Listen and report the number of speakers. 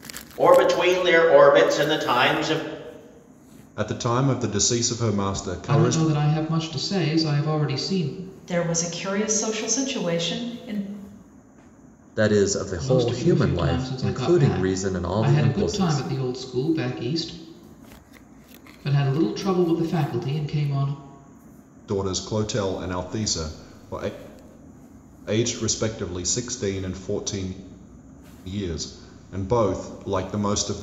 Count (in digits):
5